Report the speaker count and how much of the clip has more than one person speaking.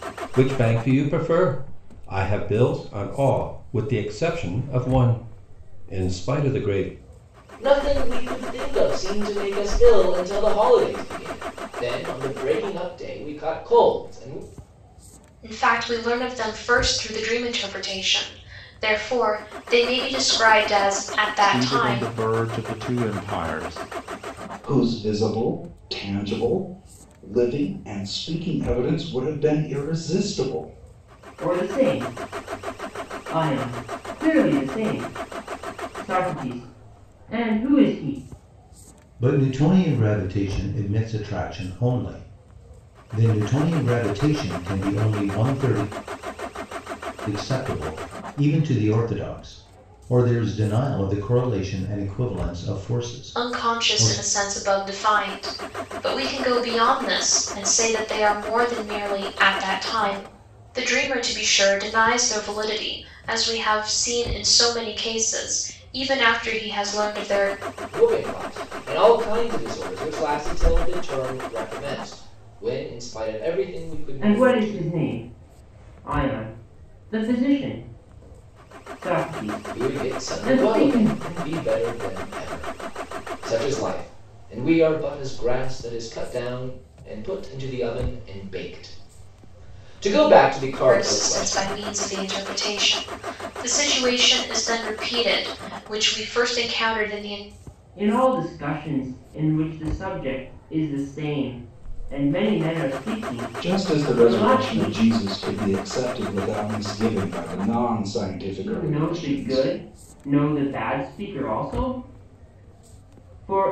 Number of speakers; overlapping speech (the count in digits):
7, about 6%